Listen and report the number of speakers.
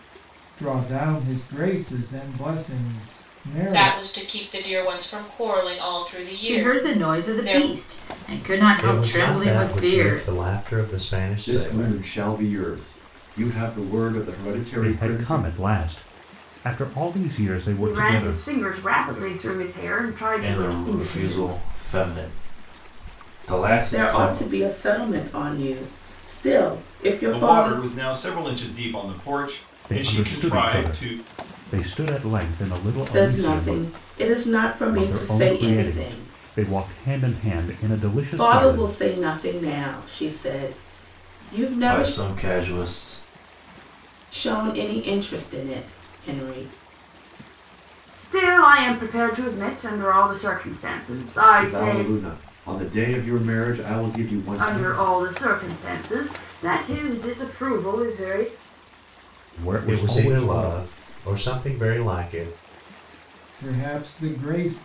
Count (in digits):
10